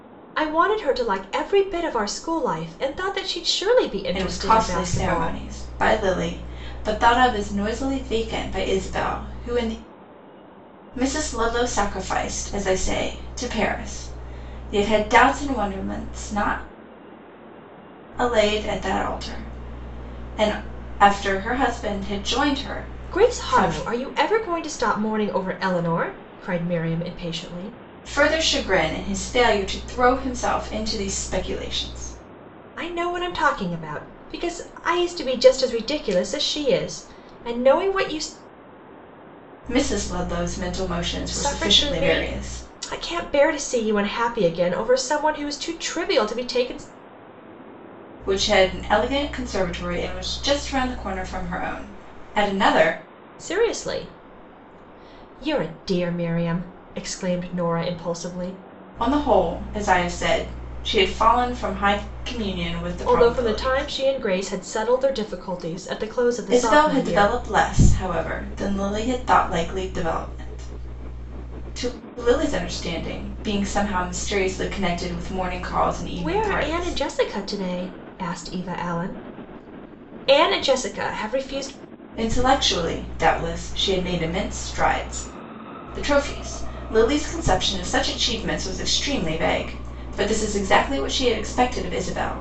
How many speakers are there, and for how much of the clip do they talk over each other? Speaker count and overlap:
2, about 6%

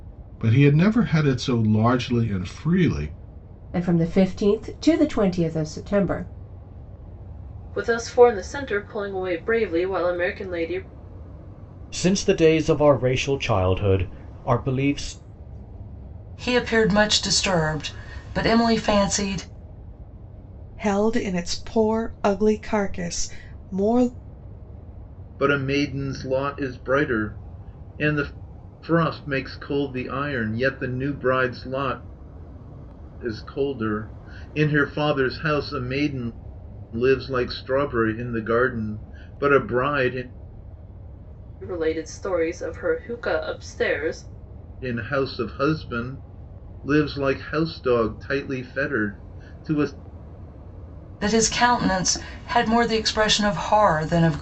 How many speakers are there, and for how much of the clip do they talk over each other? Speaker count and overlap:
7, no overlap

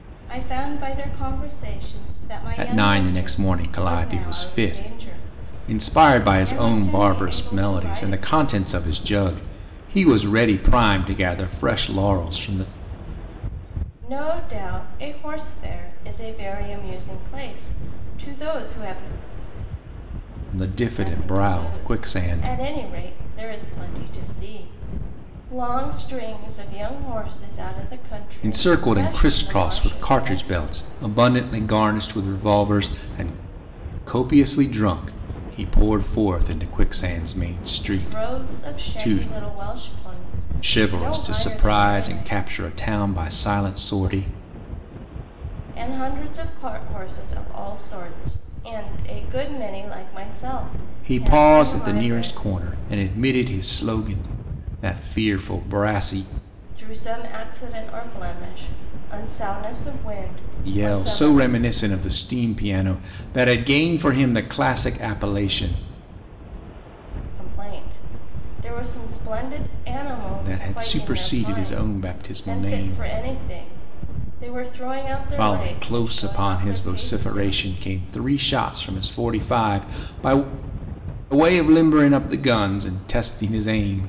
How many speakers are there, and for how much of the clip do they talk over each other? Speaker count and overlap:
2, about 22%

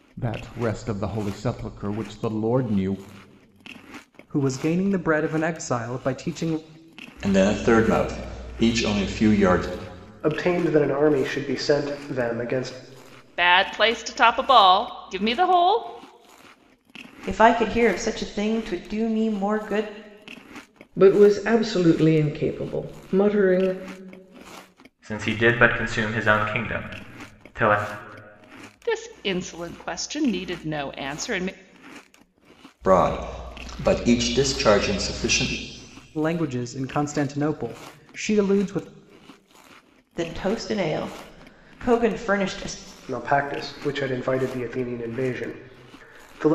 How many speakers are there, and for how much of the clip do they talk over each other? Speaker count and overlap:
8, no overlap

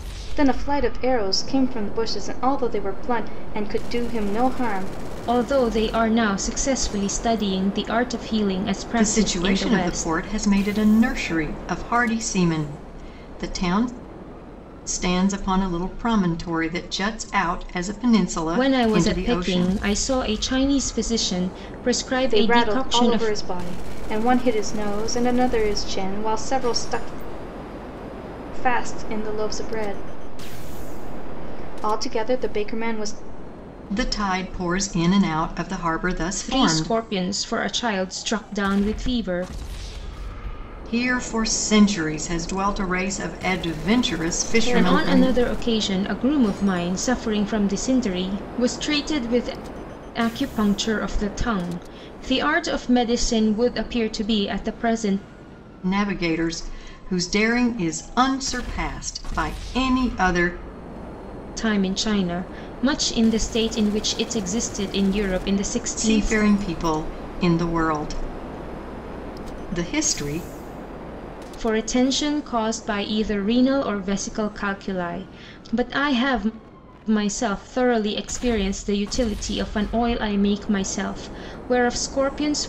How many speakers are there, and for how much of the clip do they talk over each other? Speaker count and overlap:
3, about 7%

